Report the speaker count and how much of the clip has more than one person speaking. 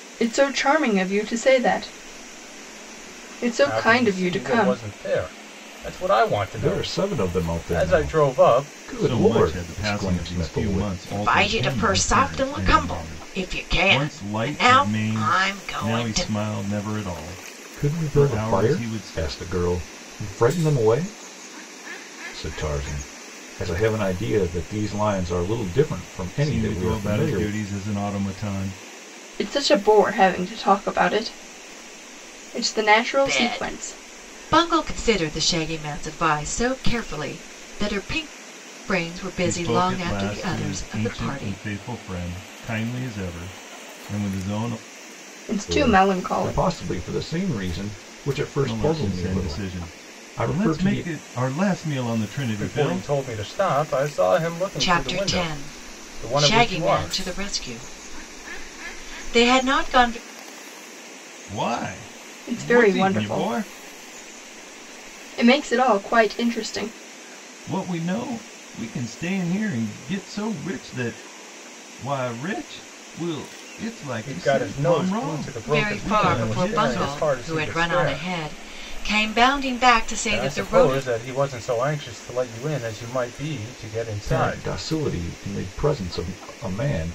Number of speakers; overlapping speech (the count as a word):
five, about 33%